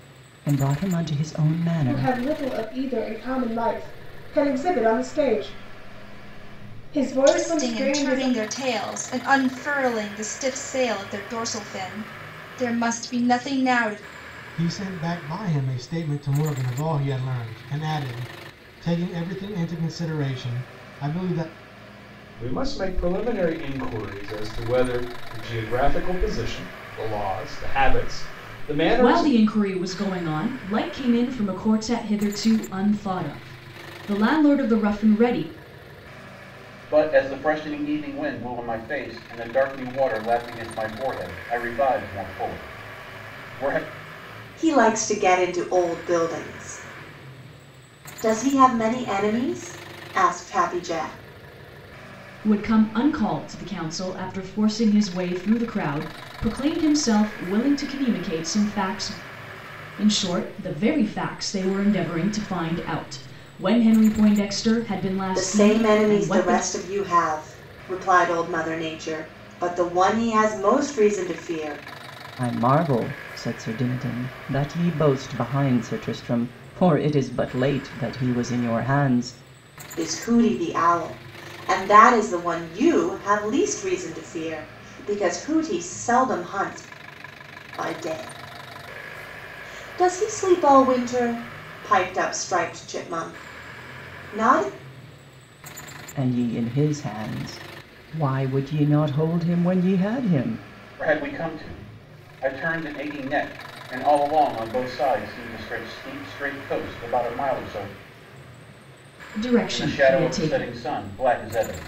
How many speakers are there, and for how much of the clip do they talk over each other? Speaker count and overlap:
eight, about 4%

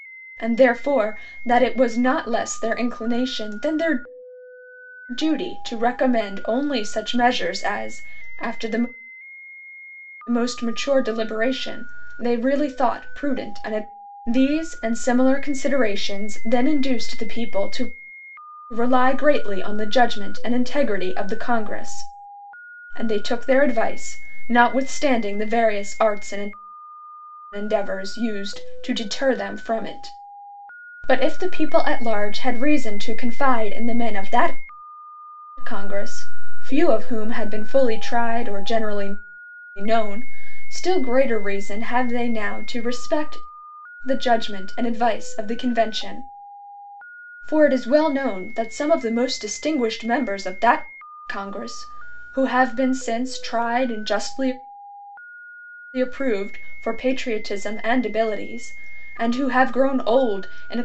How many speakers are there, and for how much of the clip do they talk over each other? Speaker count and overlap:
one, no overlap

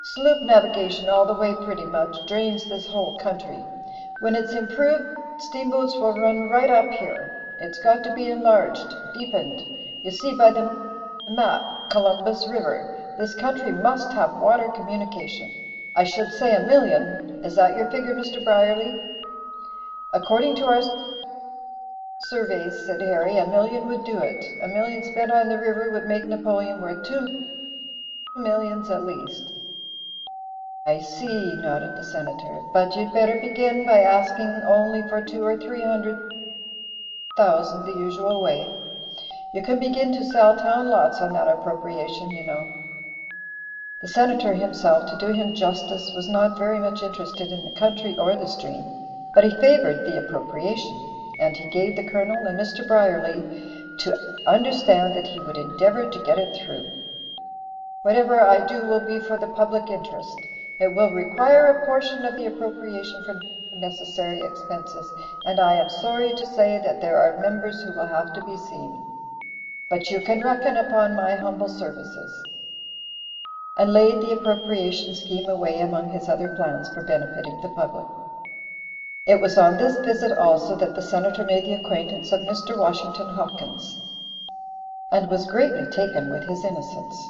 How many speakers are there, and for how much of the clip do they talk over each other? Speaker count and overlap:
one, no overlap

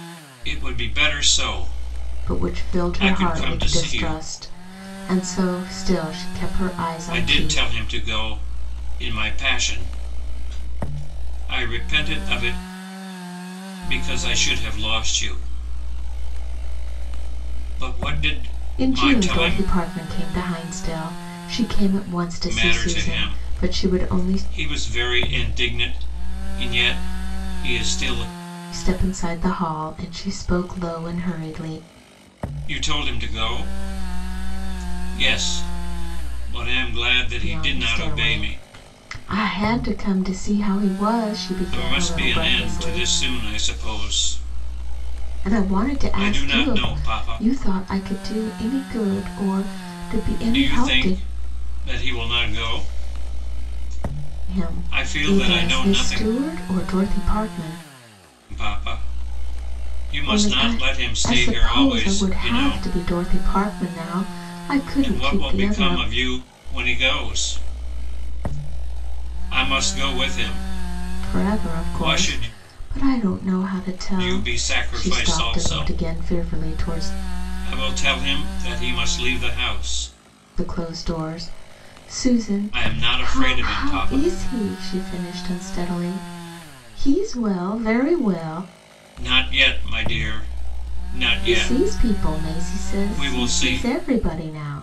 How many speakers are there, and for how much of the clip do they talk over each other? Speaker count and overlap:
two, about 26%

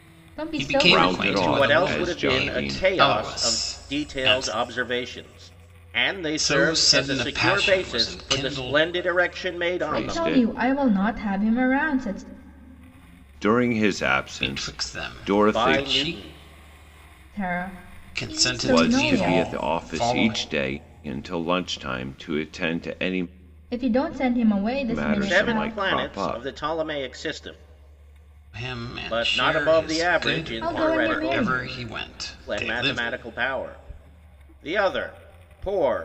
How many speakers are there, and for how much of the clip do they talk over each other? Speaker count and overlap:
four, about 45%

